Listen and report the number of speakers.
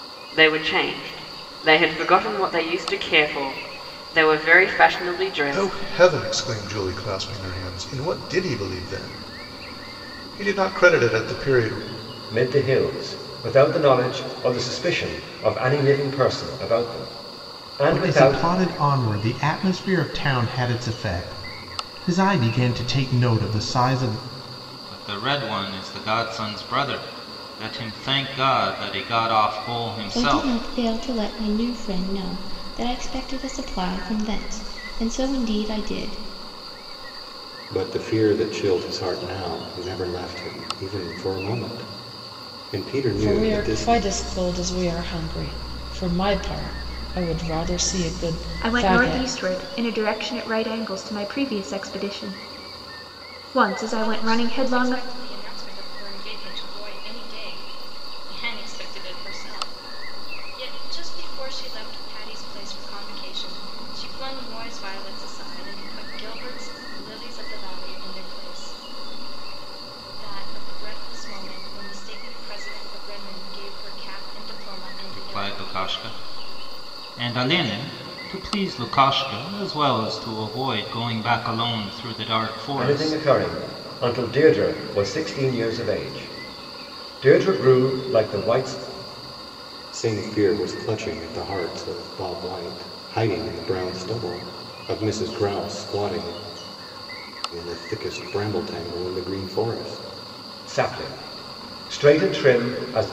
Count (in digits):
10